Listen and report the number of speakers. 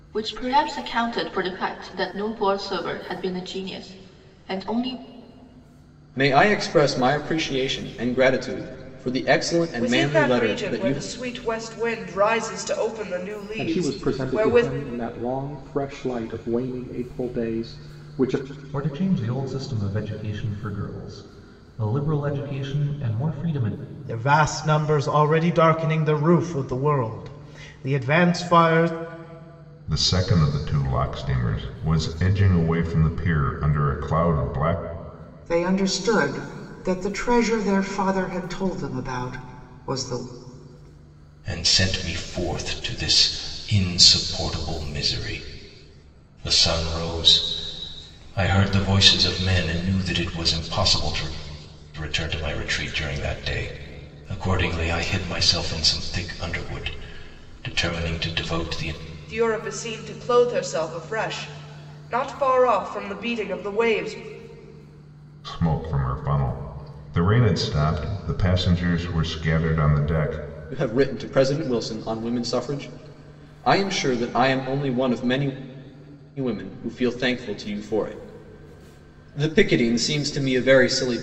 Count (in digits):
9